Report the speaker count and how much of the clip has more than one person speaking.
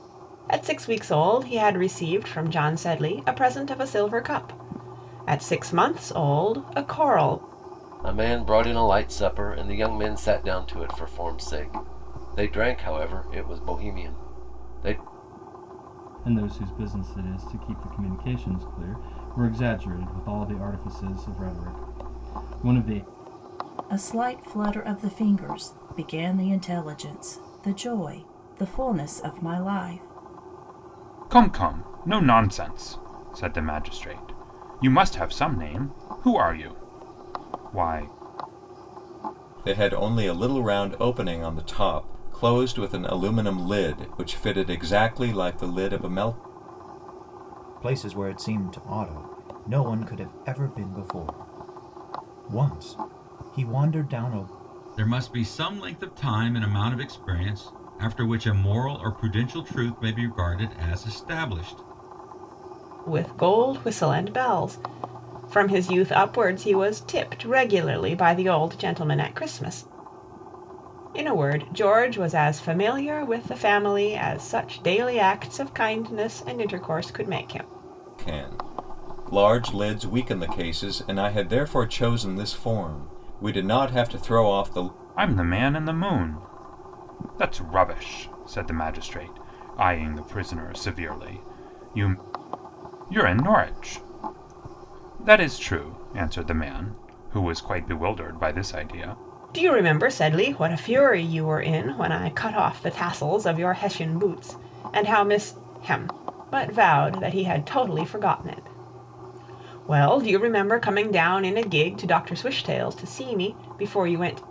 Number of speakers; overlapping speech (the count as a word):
eight, no overlap